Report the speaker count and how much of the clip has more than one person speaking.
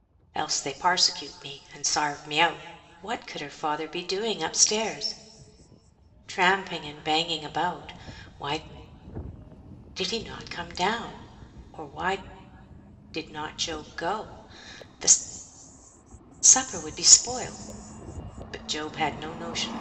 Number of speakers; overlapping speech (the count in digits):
1, no overlap